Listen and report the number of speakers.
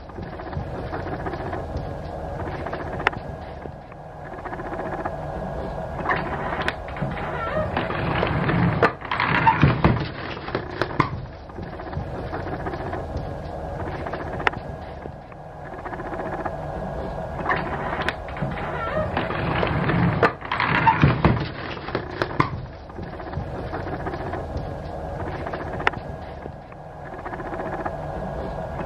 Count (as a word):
zero